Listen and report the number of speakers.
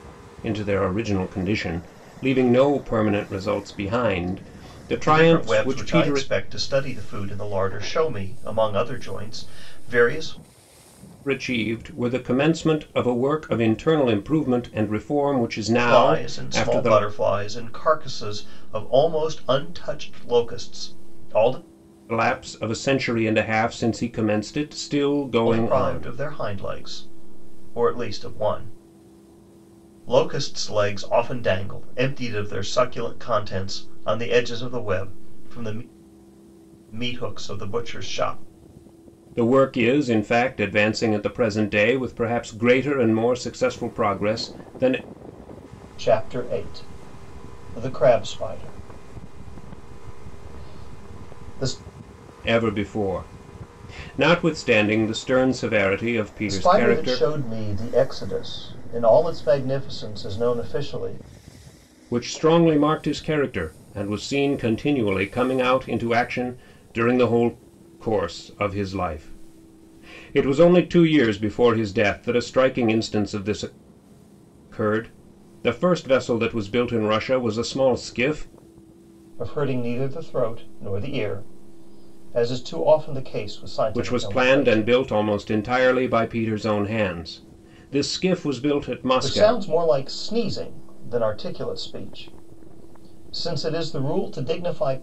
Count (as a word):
two